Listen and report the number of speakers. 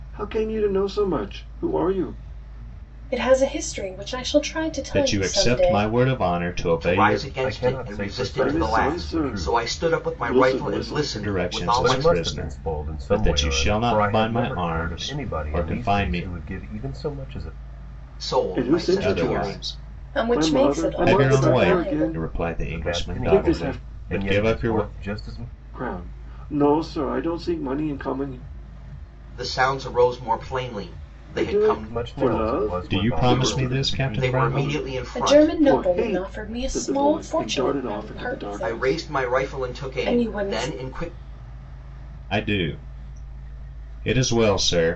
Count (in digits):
5